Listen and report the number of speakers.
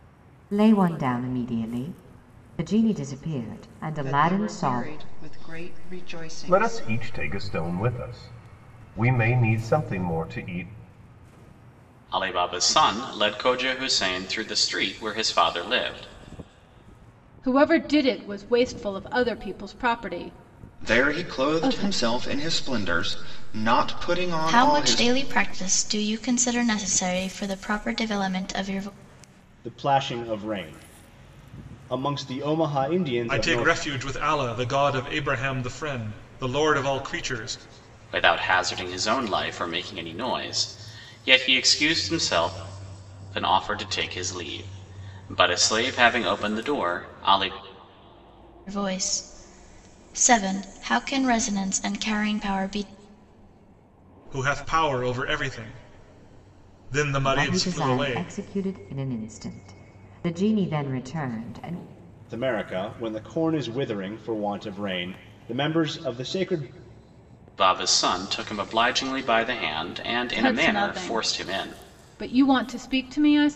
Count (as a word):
nine